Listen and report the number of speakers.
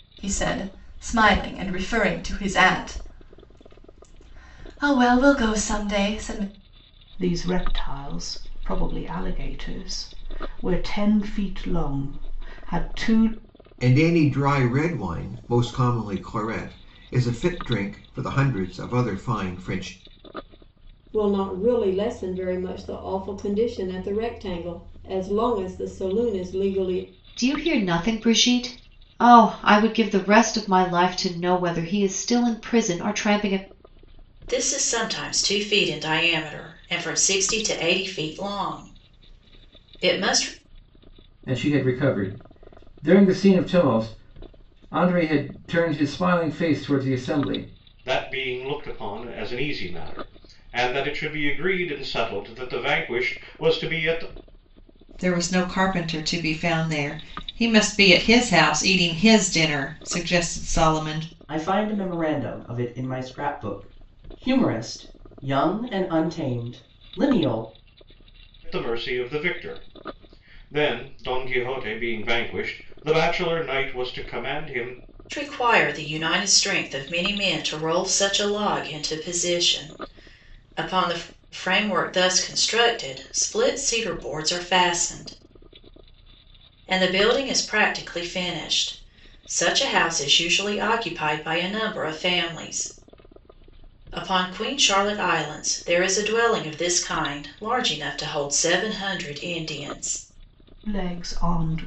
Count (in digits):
10